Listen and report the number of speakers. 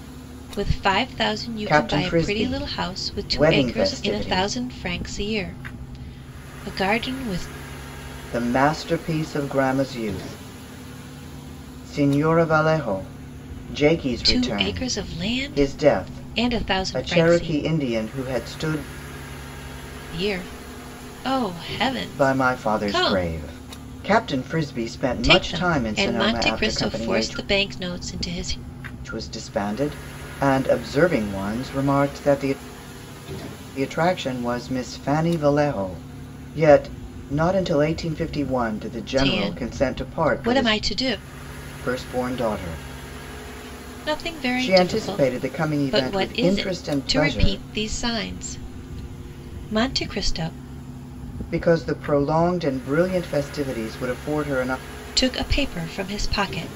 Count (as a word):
two